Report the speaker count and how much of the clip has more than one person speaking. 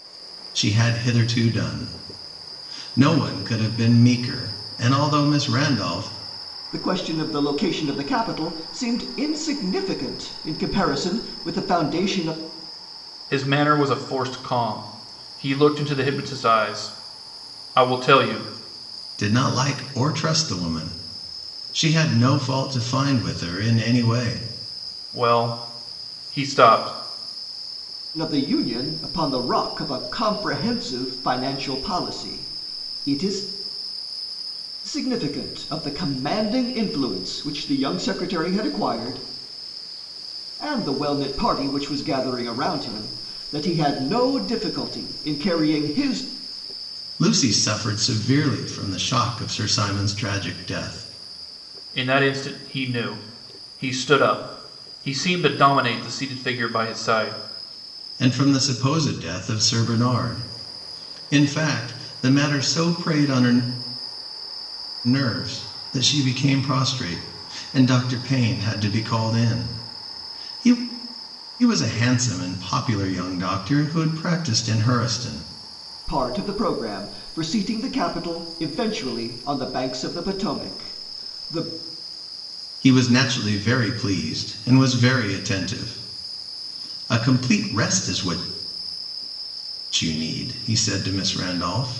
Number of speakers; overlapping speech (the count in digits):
3, no overlap